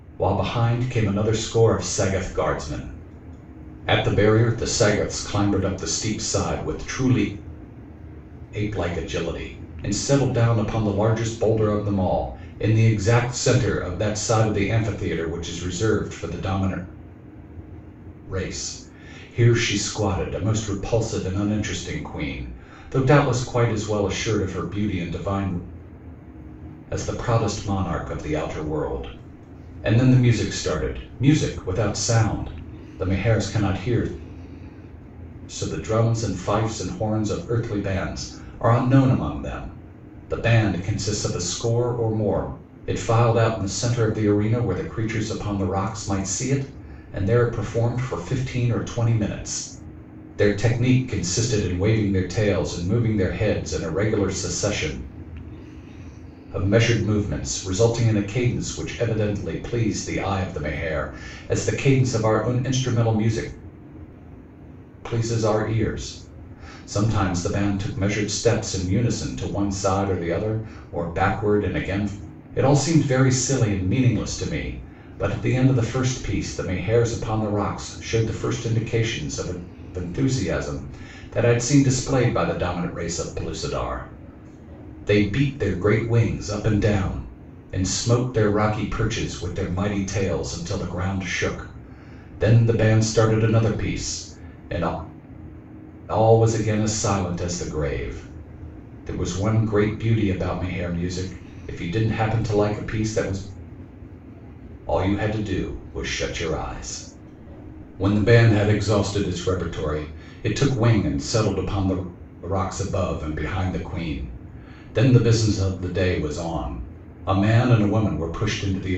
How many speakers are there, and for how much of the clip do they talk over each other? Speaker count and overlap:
1, no overlap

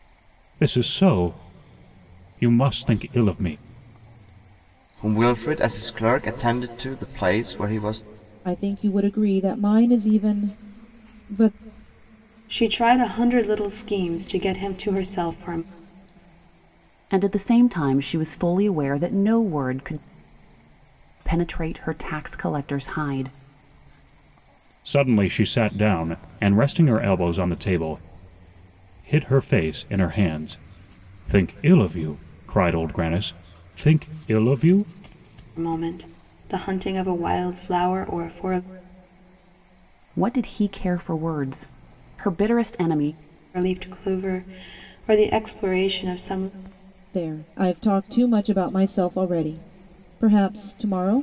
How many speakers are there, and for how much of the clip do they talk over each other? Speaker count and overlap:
5, no overlap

